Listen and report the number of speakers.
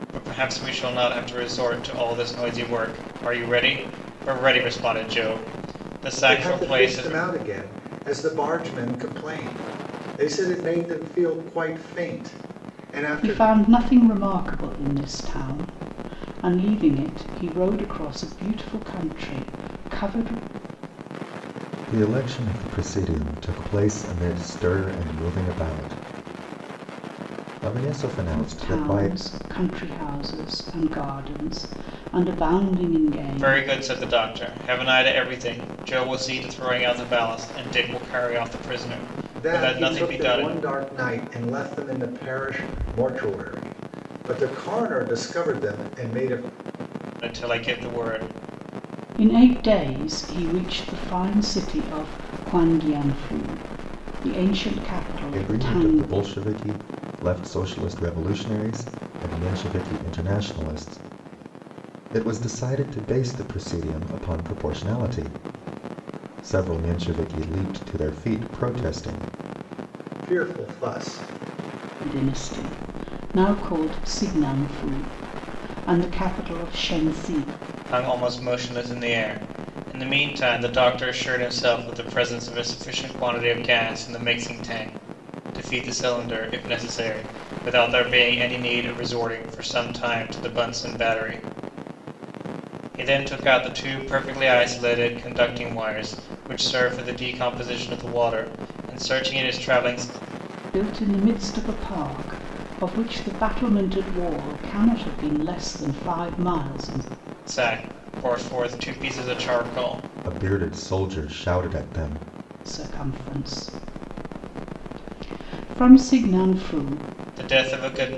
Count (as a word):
four